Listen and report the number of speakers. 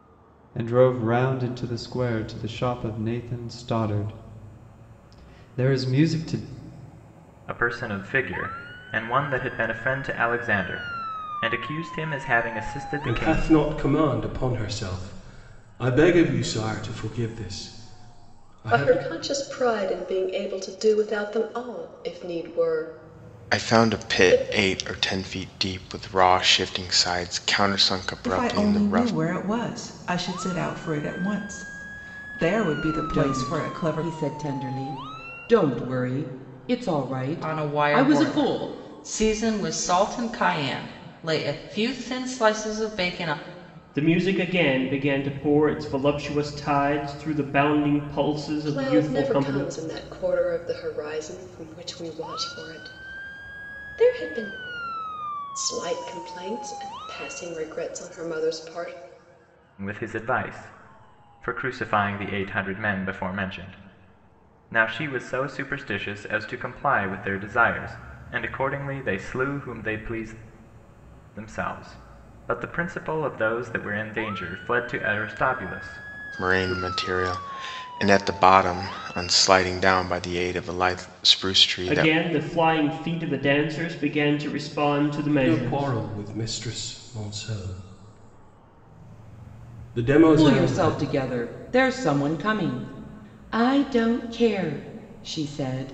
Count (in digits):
9